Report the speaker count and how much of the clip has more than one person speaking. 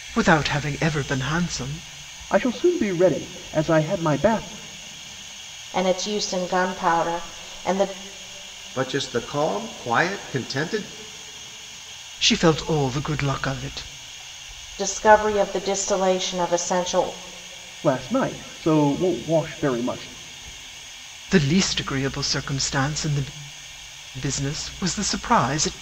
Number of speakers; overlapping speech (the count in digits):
4, no overlap